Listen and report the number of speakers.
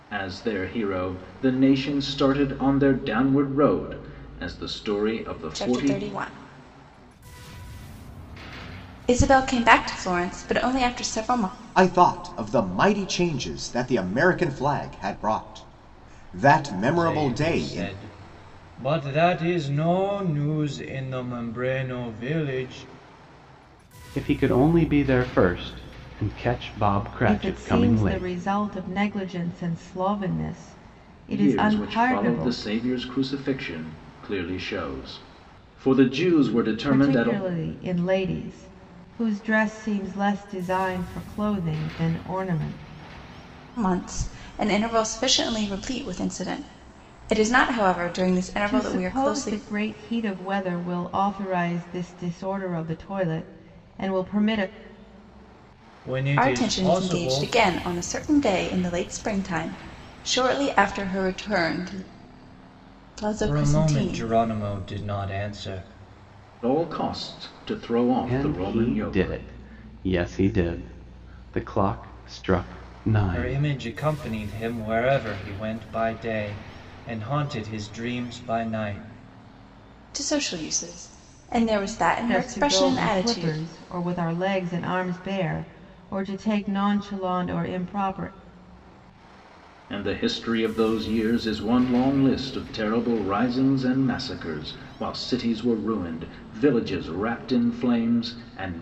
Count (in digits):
6